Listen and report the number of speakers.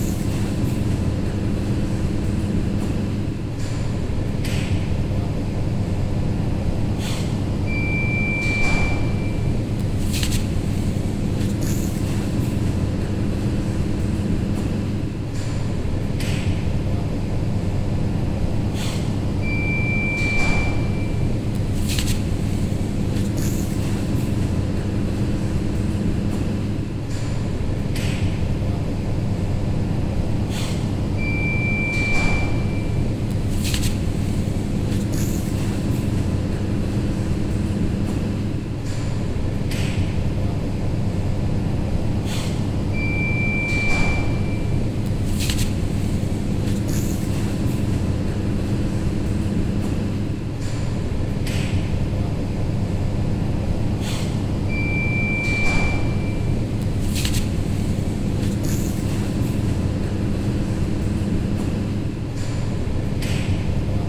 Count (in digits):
0